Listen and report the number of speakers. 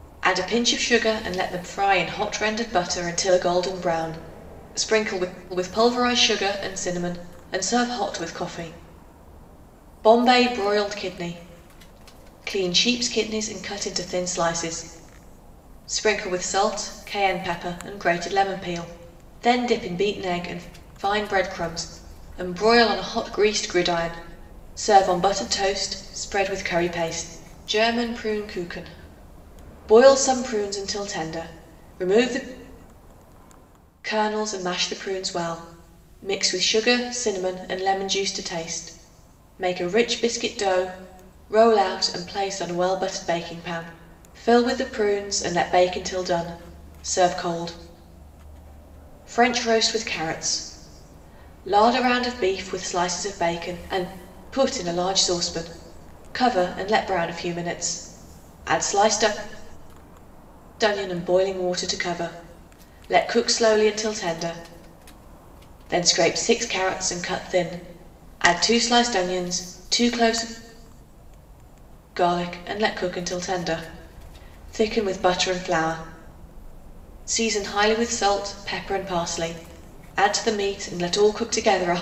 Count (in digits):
1